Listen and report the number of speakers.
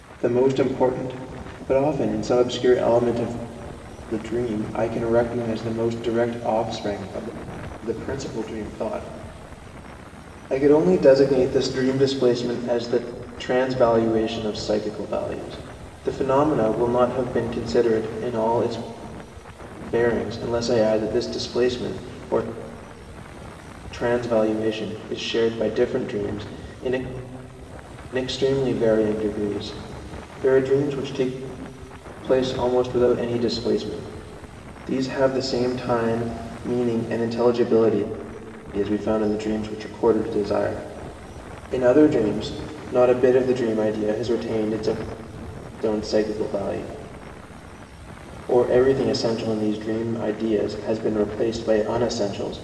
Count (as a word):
one